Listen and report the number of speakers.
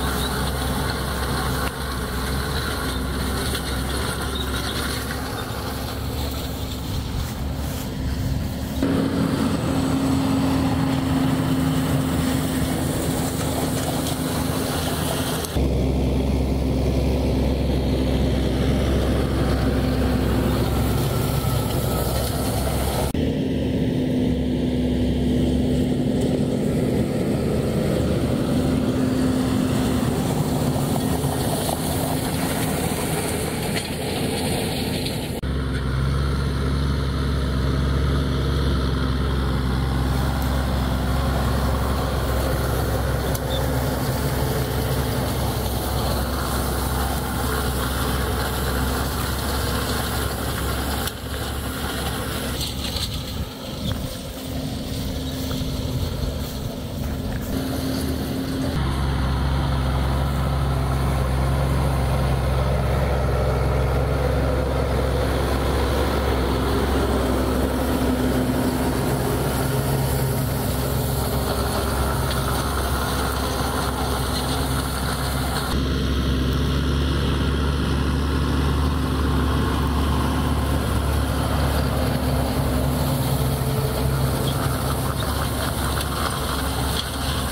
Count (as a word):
zero